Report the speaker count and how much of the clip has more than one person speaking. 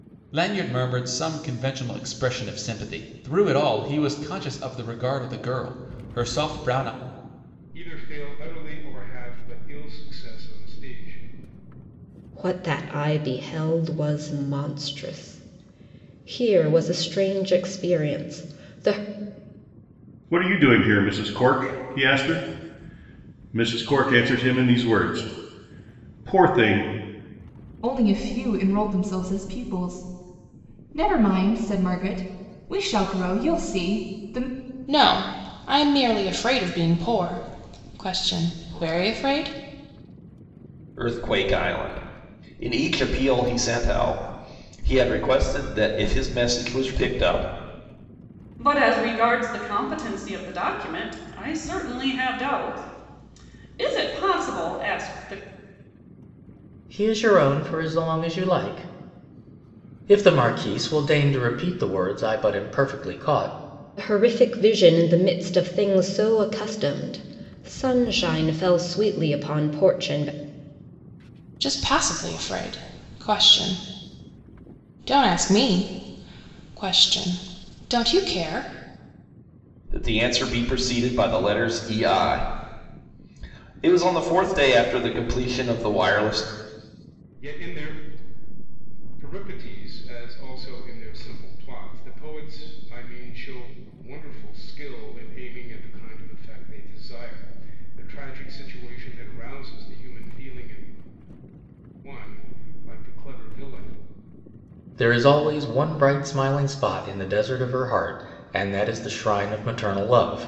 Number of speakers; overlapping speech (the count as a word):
nine, no overlap